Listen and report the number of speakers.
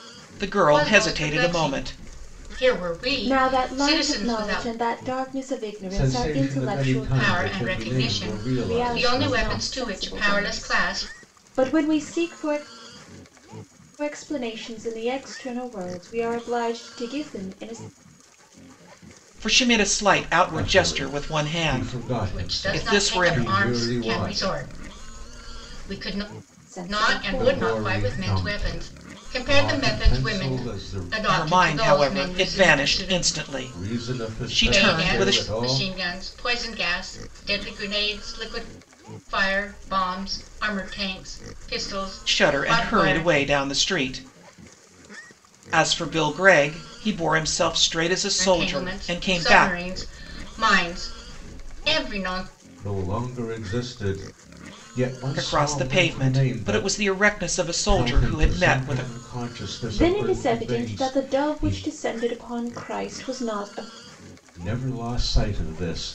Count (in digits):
4